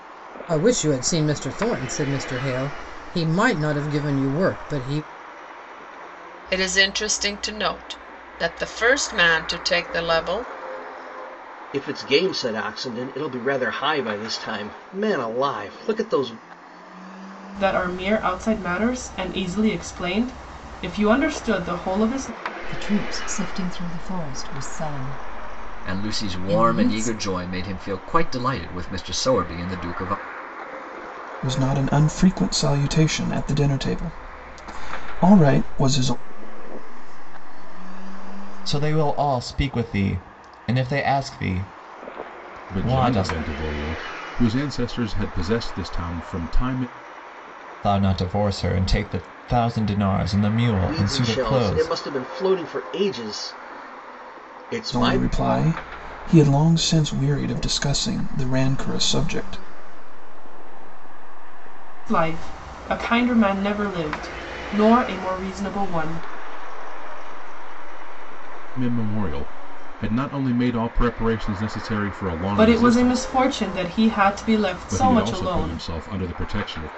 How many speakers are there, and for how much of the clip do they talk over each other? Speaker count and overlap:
ten, about 14%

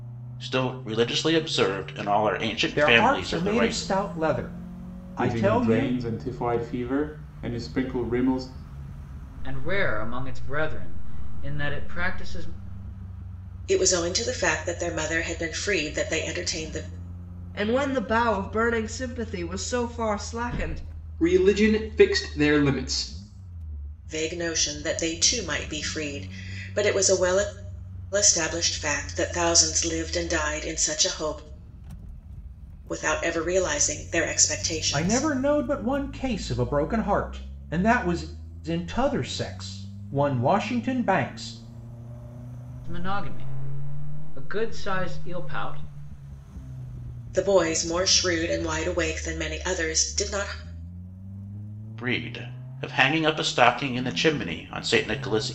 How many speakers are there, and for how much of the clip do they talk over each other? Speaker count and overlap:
seven, about 4%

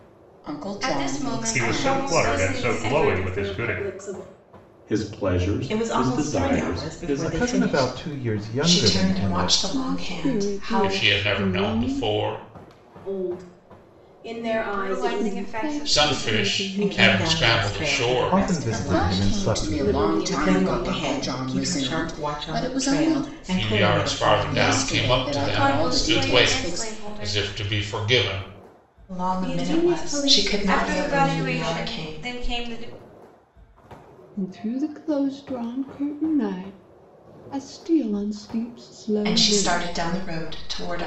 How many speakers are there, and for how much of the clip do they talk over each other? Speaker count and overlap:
ten, about 61%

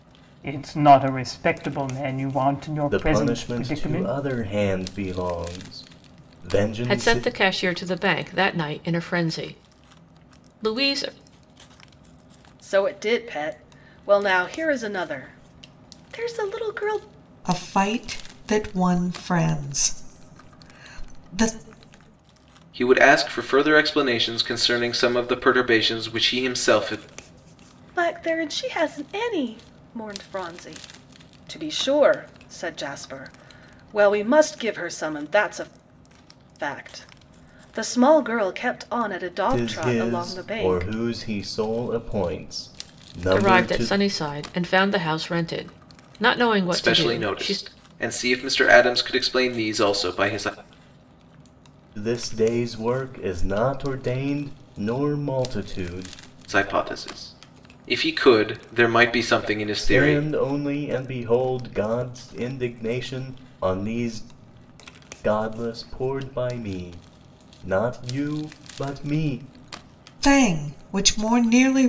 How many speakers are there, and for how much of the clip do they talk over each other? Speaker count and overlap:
six, about 7%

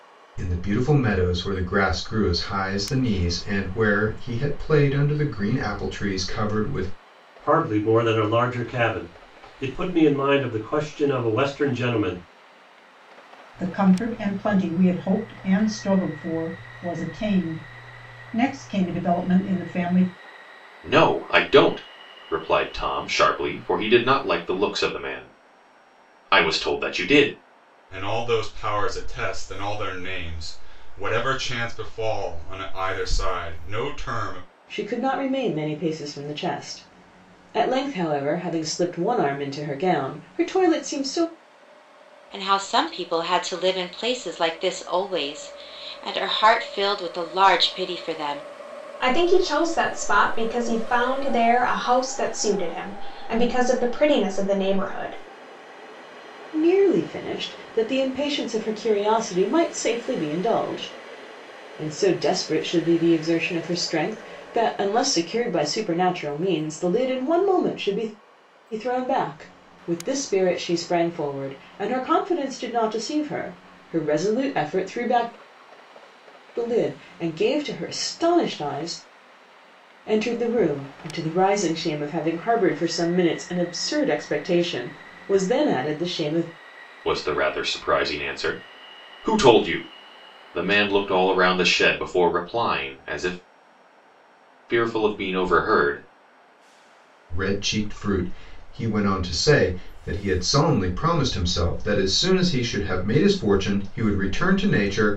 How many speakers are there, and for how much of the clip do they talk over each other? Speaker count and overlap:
eight, no overlap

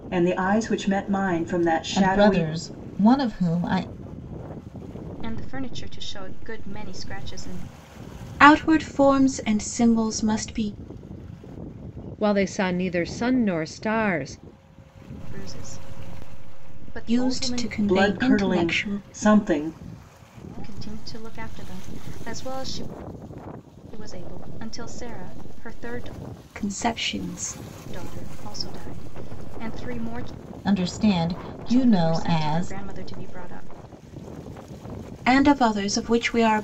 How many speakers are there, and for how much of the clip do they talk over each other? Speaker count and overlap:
five, about 10%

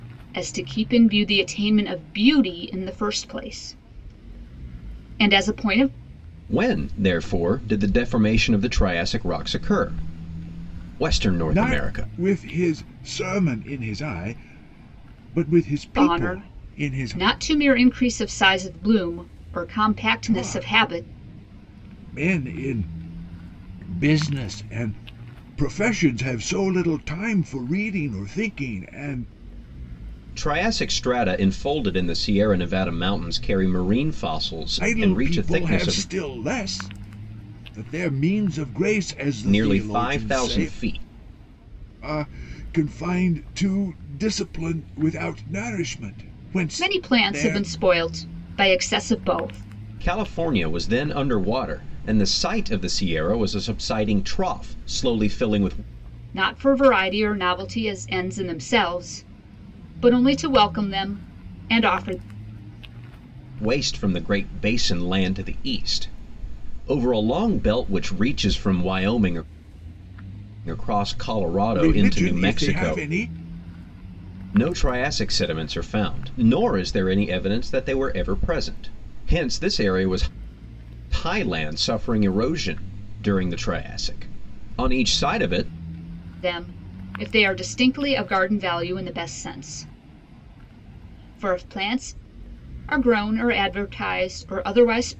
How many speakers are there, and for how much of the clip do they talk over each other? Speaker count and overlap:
three, about 8%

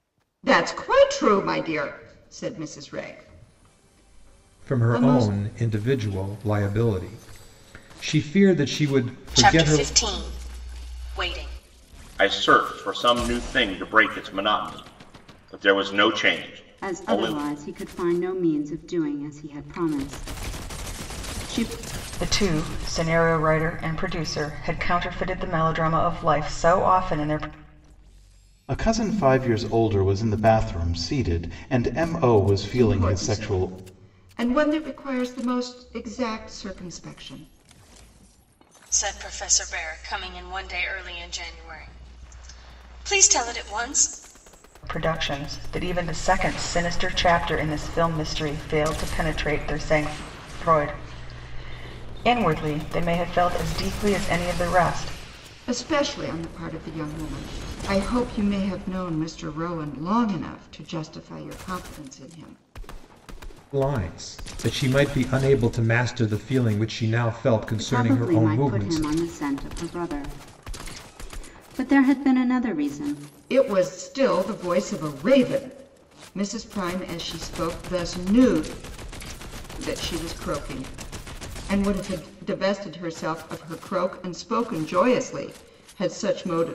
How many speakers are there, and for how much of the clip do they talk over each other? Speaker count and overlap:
seven, about 5%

